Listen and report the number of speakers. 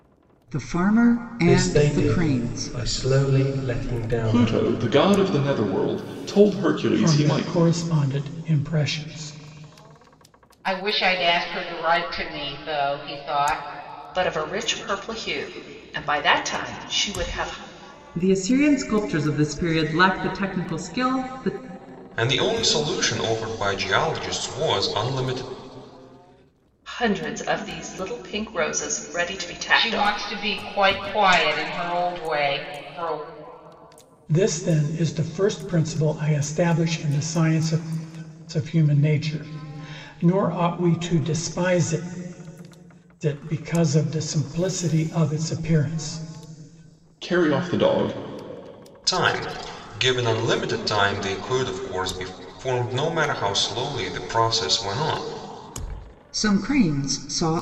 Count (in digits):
8